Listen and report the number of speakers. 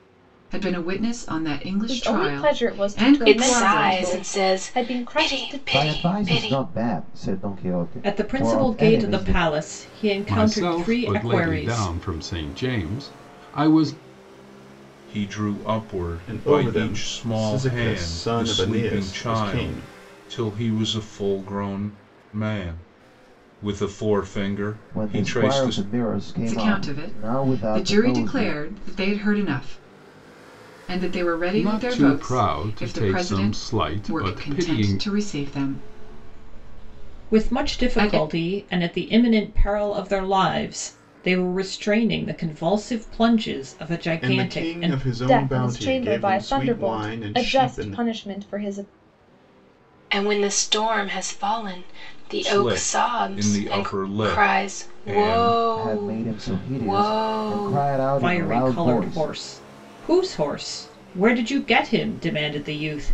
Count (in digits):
8